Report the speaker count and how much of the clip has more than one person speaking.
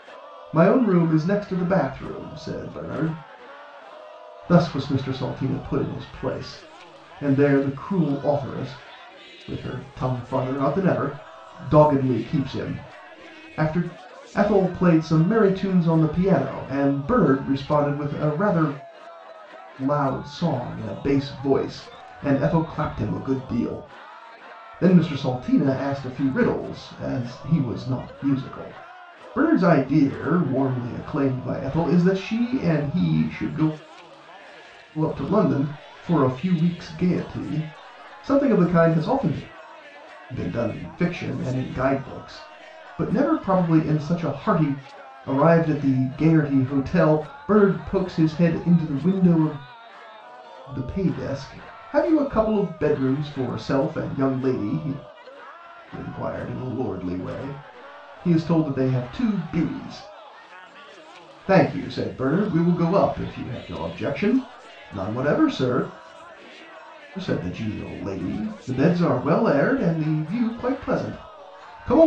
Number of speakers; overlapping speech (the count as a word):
one, no overlap